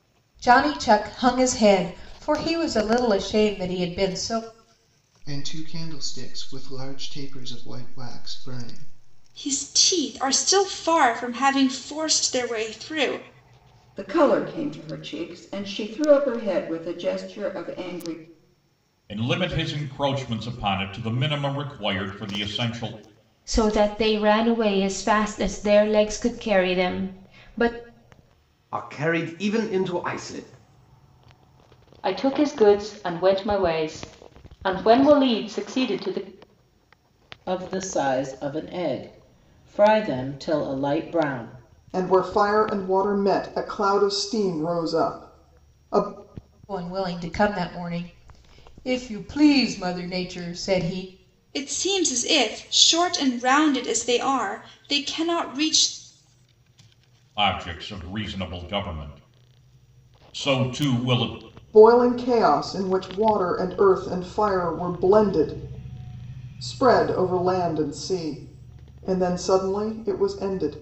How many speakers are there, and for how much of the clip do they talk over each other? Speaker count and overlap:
ten, no overlap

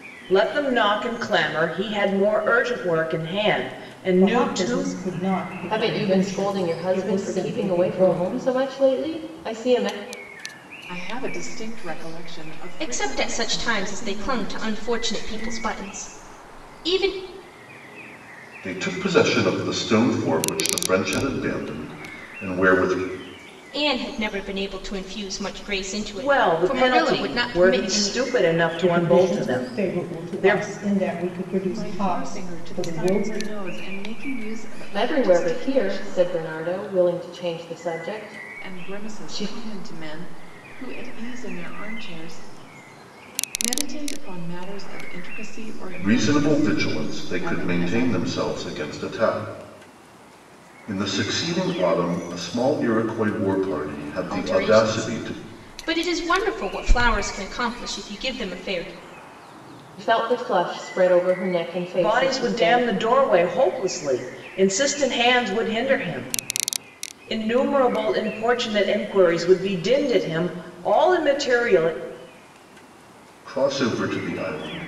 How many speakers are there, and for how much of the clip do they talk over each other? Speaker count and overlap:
six, about 25%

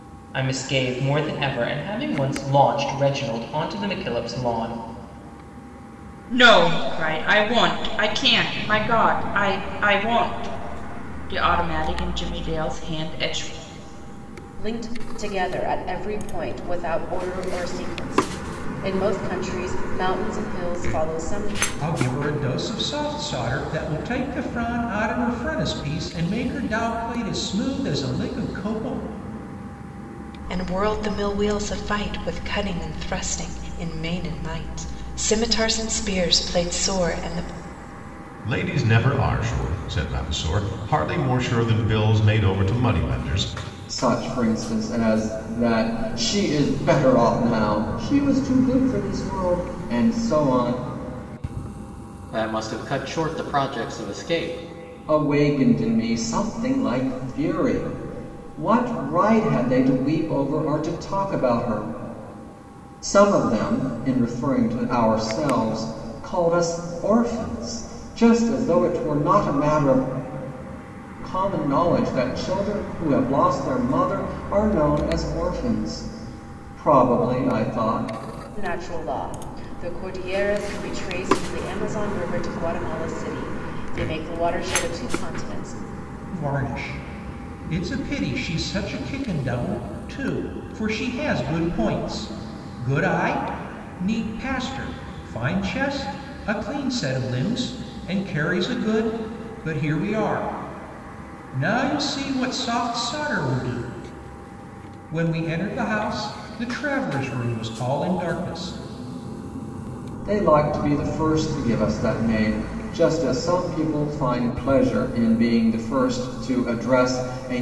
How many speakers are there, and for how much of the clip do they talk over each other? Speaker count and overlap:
eight, no overlap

